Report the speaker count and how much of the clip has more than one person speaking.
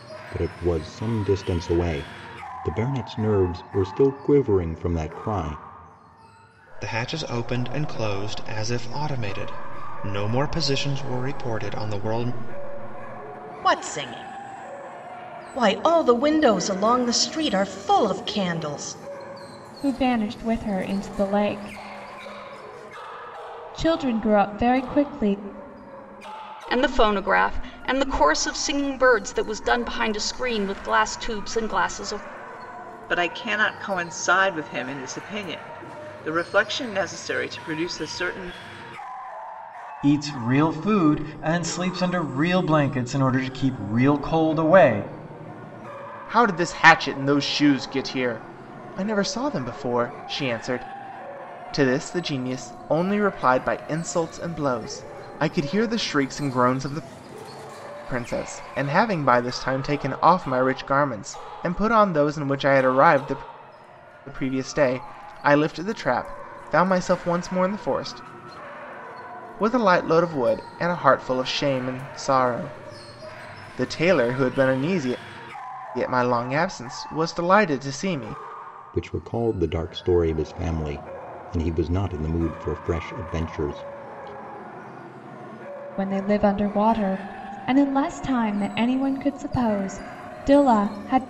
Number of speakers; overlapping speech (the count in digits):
8, no overlap